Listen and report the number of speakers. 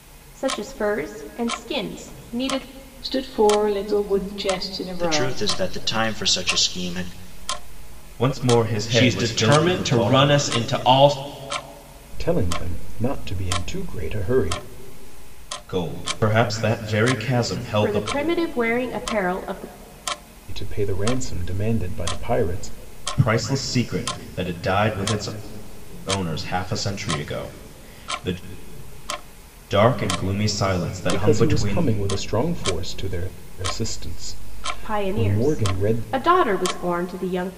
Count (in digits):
6